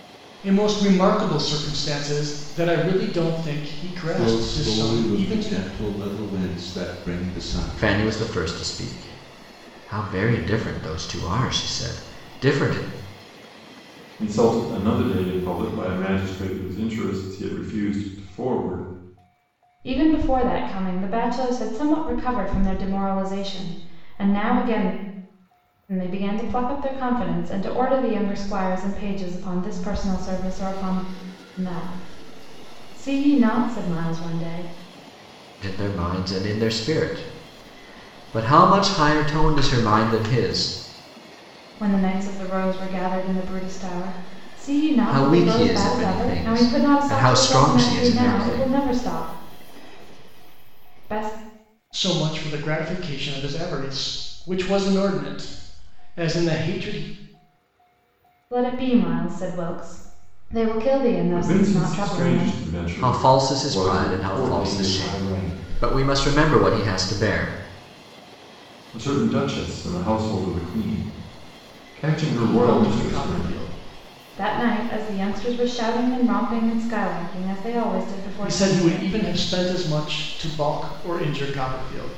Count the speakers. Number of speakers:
5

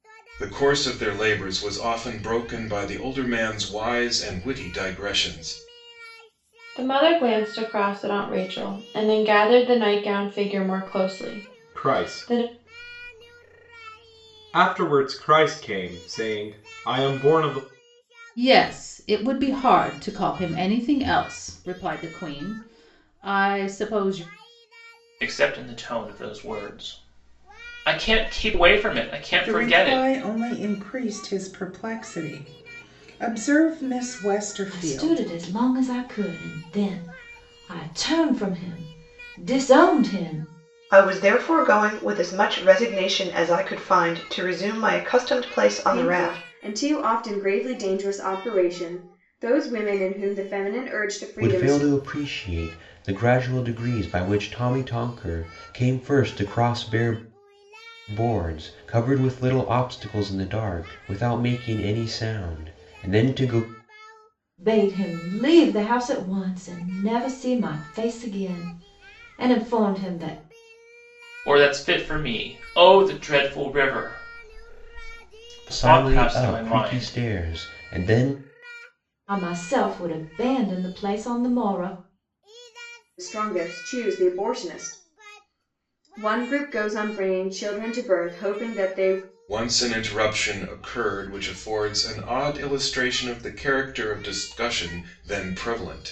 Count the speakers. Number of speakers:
10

